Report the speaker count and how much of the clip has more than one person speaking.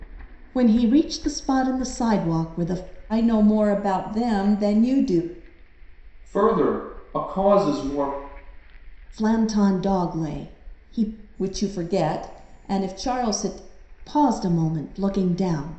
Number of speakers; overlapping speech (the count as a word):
three, no overlap